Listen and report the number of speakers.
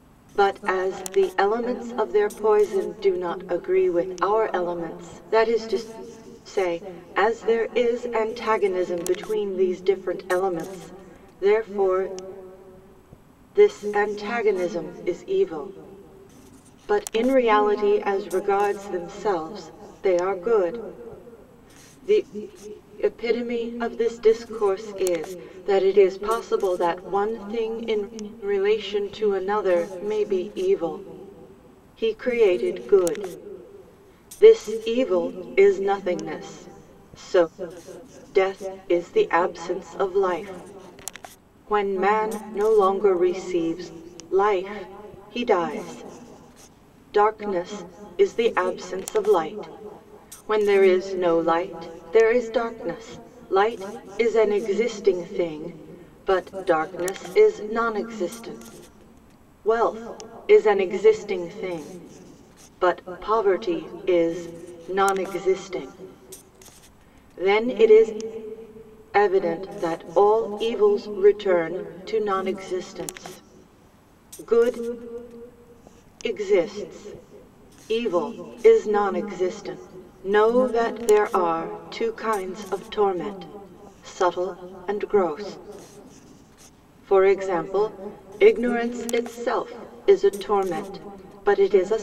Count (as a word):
one